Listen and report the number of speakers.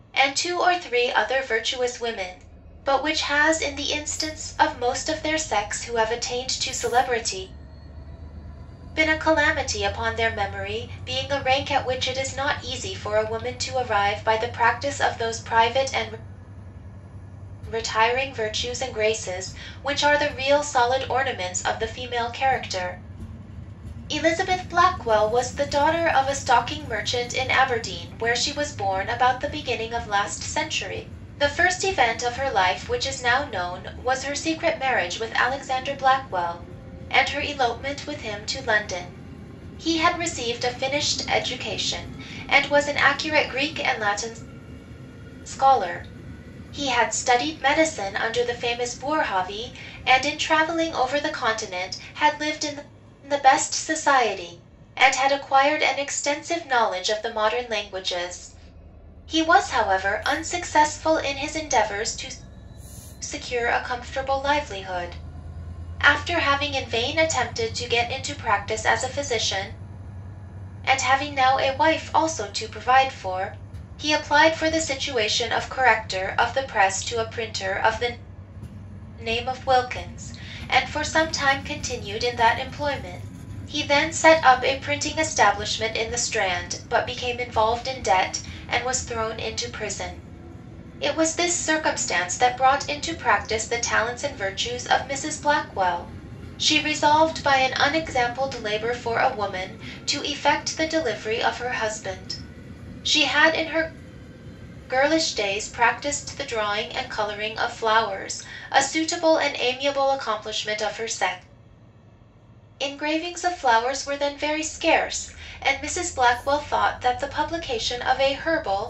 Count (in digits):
1